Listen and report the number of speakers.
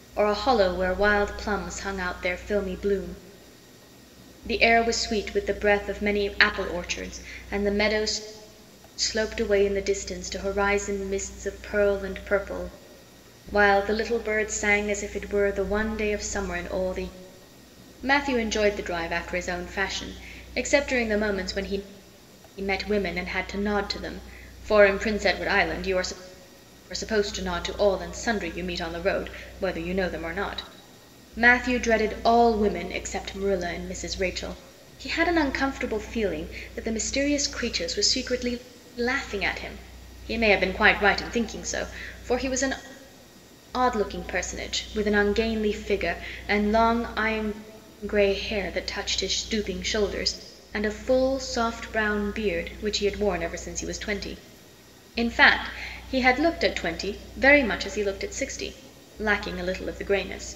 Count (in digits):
1